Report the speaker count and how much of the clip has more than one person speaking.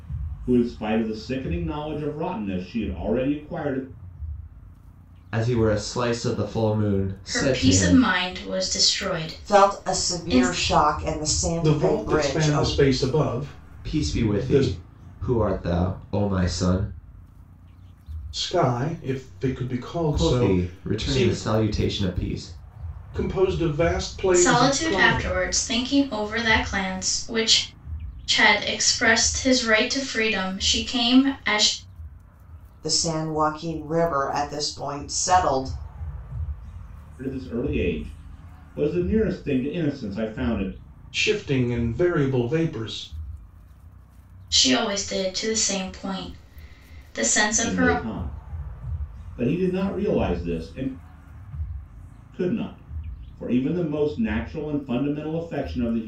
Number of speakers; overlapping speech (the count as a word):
five, about 12%